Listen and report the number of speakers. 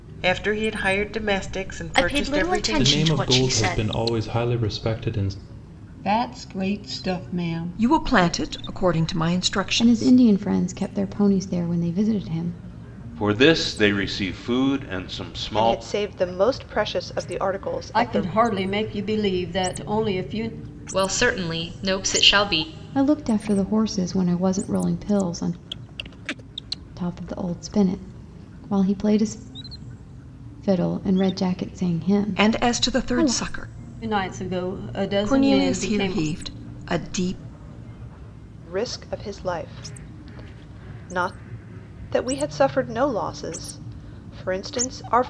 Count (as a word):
ten